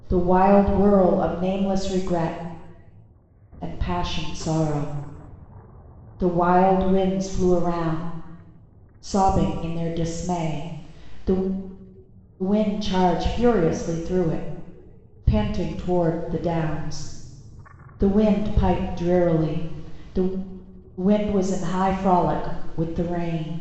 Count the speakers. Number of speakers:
1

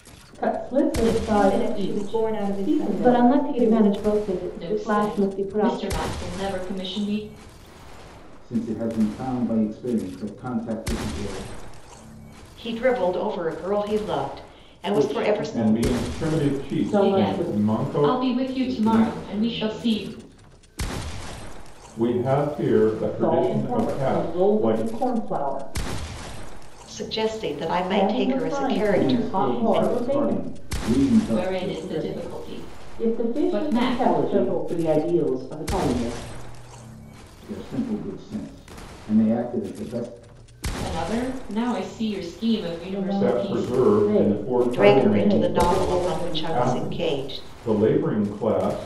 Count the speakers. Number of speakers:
8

